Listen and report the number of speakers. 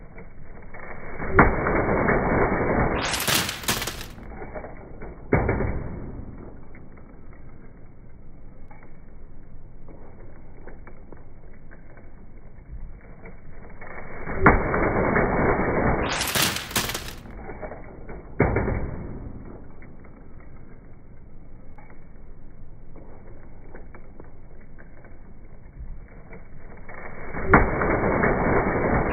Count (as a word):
zero